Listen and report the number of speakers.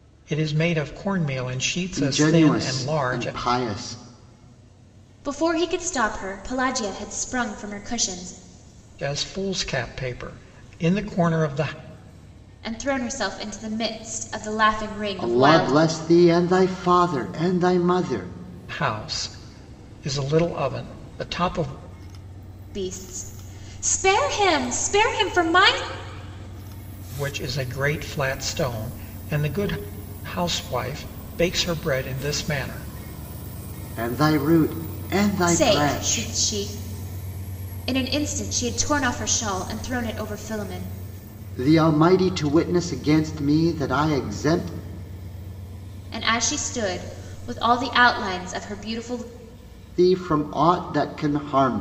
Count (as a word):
three